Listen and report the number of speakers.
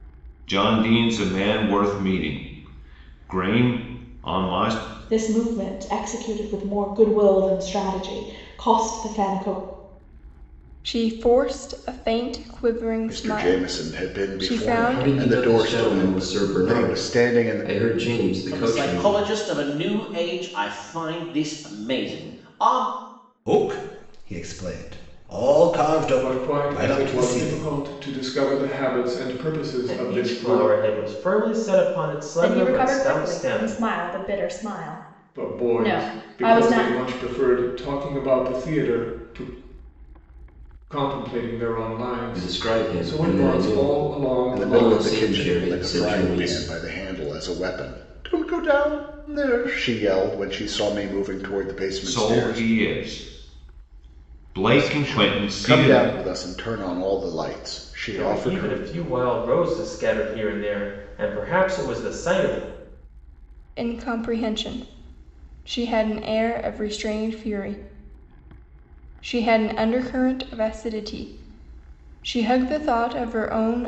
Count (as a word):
ten